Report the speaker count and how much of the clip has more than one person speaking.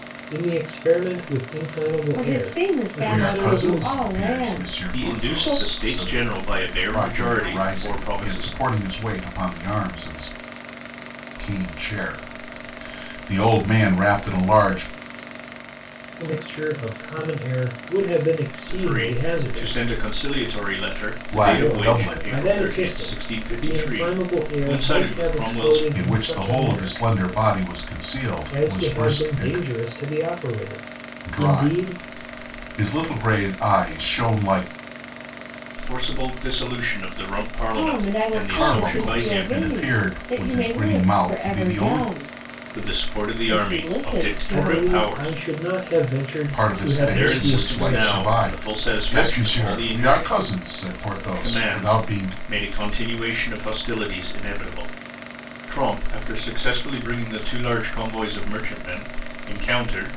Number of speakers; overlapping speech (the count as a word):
four, about 44%